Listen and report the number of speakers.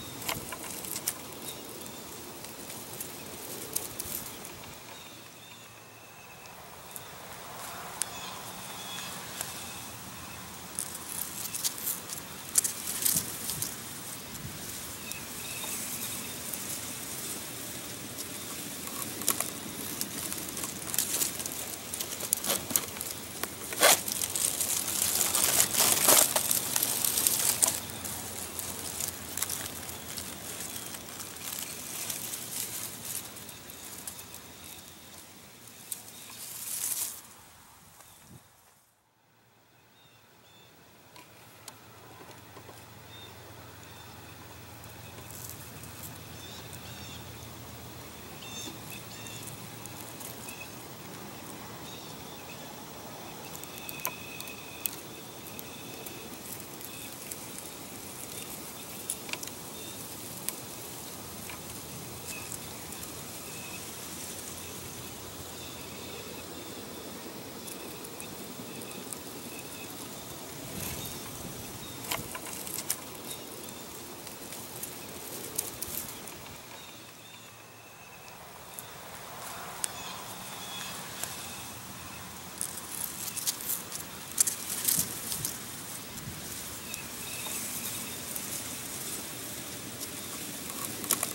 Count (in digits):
0